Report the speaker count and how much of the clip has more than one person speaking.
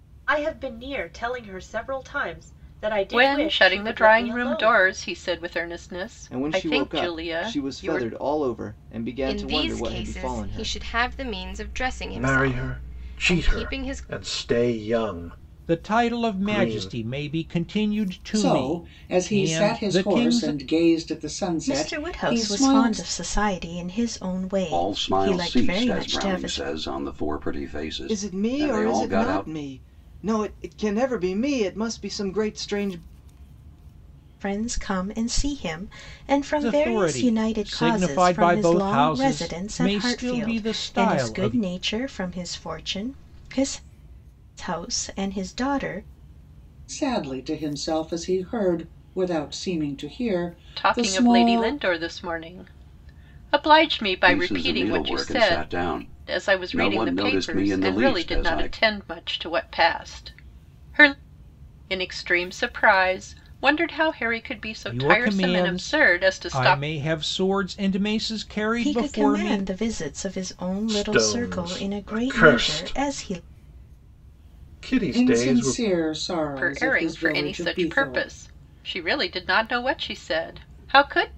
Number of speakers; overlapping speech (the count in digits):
9, about 41%